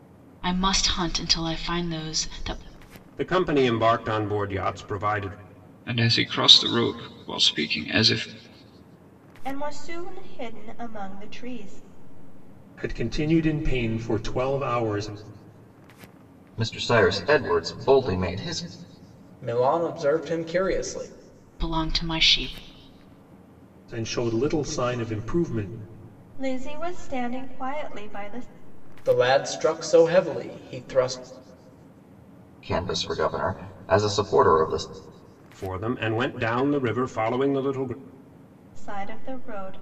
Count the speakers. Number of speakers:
7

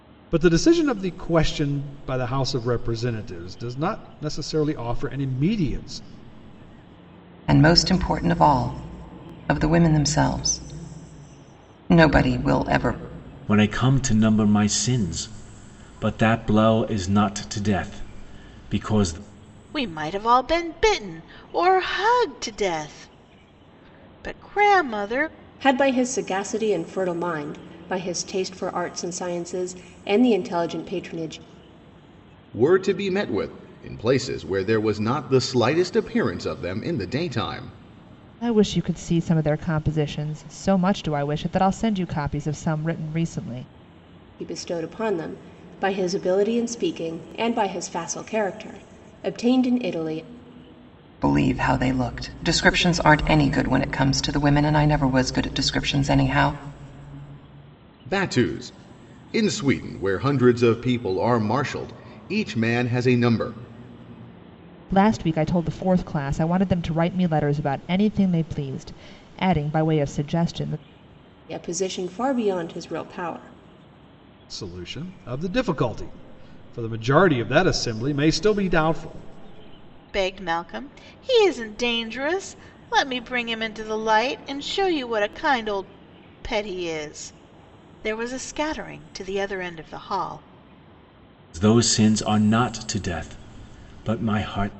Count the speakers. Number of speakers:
7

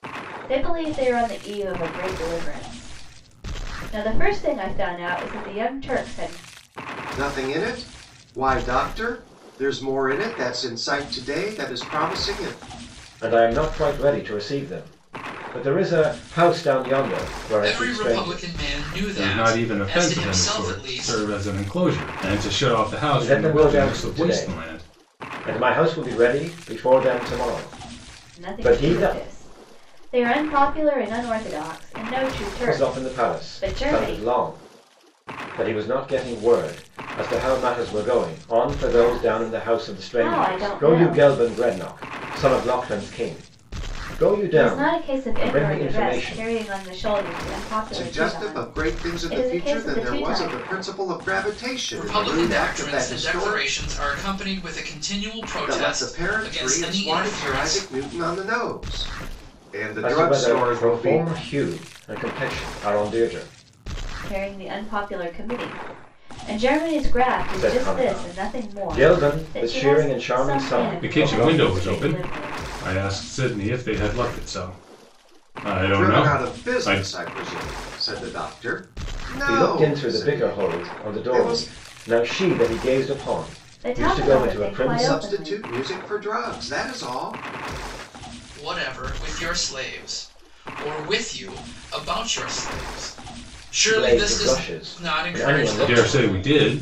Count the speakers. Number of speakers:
5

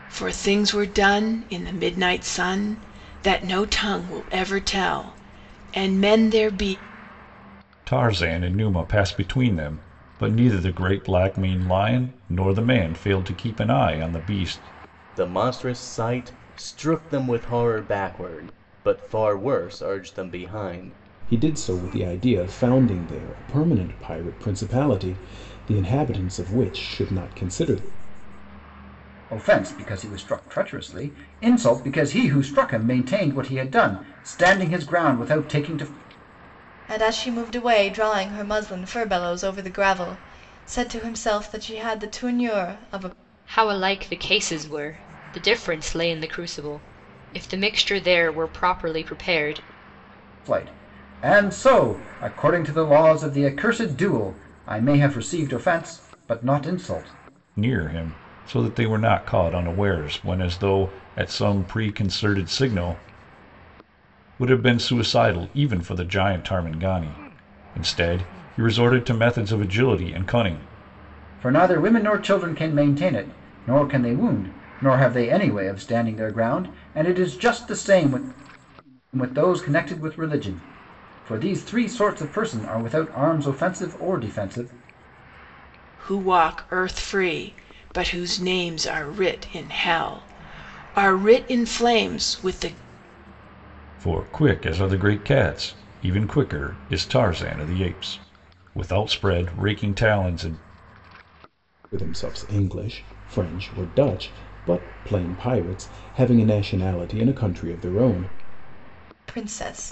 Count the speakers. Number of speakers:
7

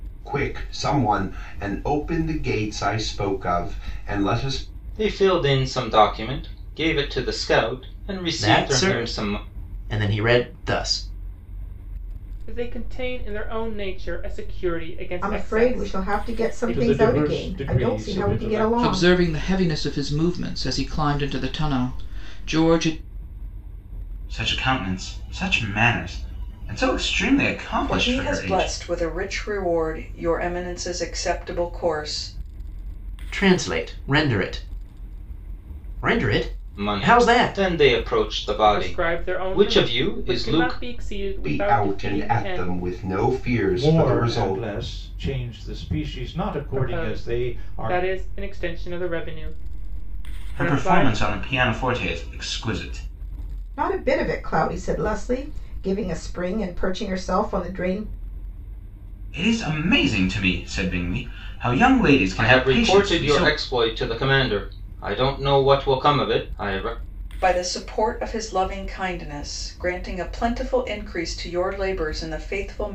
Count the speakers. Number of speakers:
9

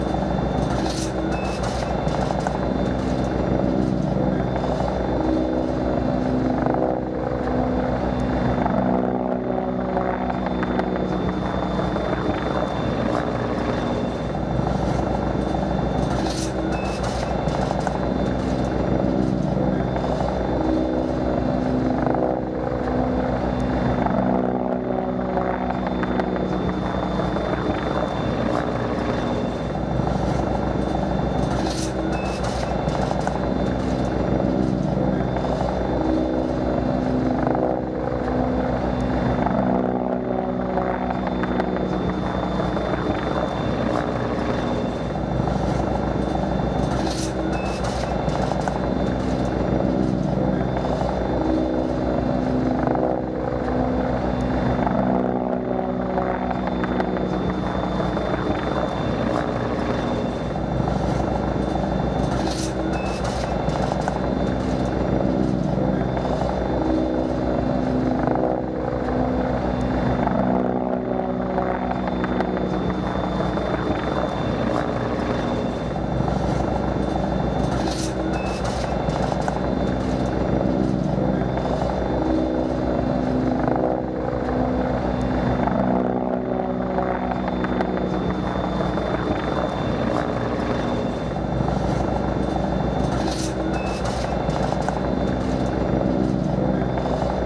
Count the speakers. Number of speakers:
0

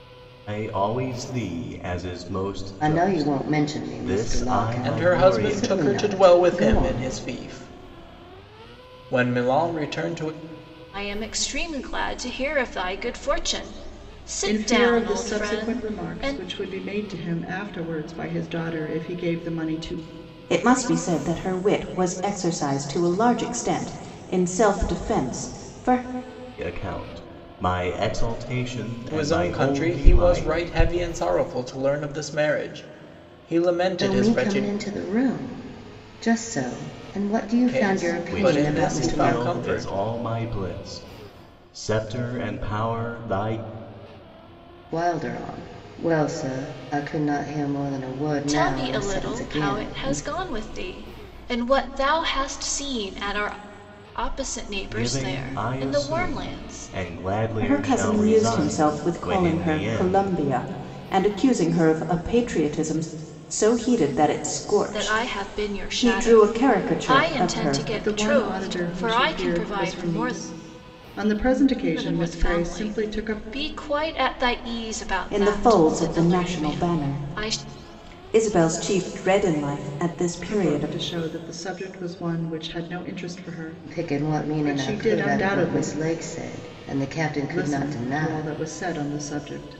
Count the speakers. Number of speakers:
6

